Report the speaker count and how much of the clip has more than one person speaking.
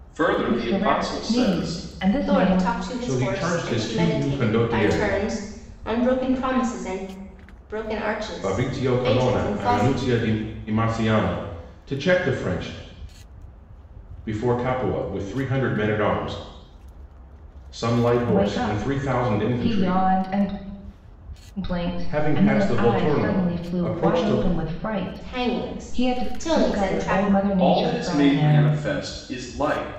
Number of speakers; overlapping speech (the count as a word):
four, about 43%